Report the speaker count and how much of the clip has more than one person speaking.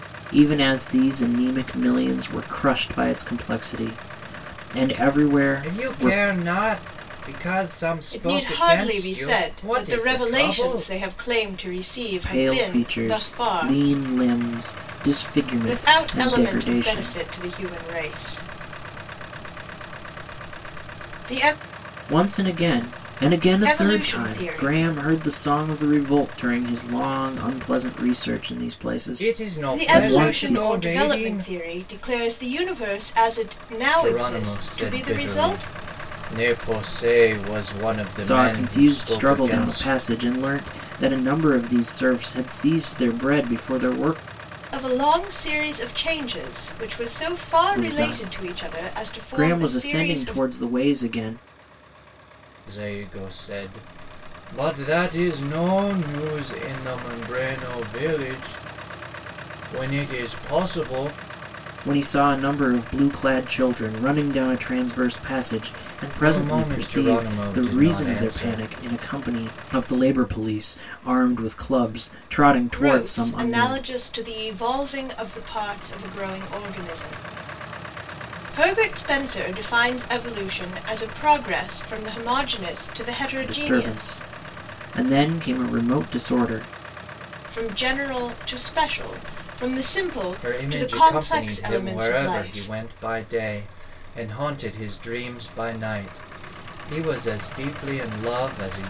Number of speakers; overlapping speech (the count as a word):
three, about 23%